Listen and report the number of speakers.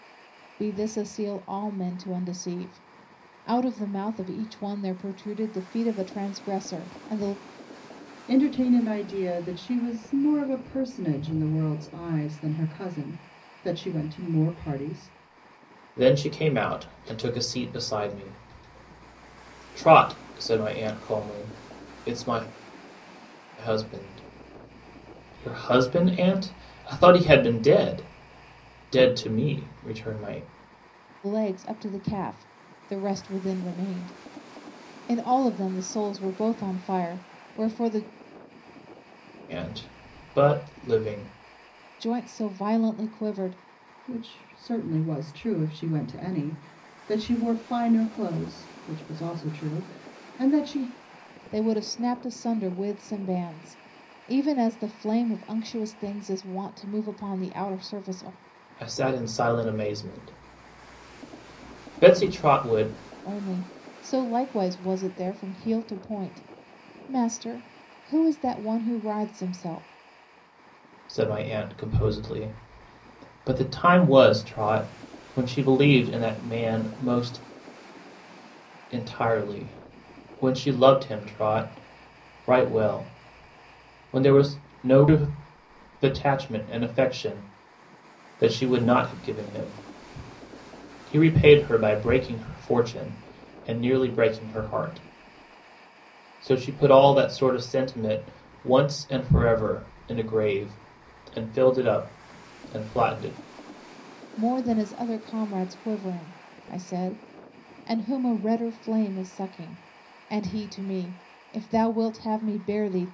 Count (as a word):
three